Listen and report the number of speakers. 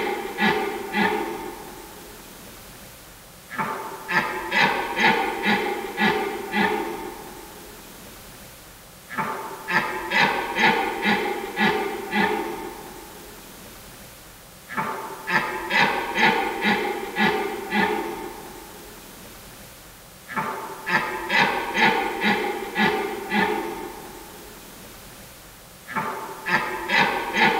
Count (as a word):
zero